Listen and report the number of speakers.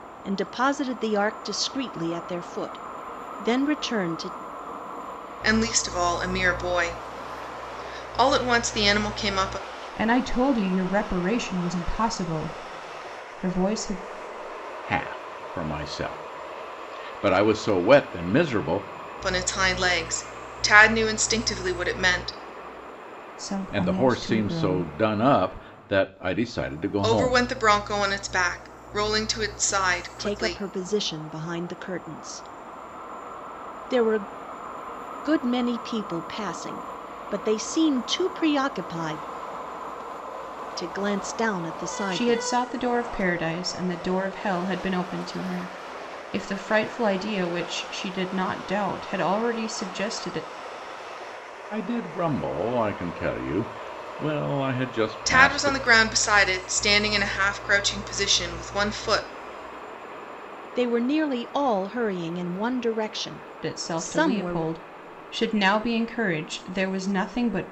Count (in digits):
4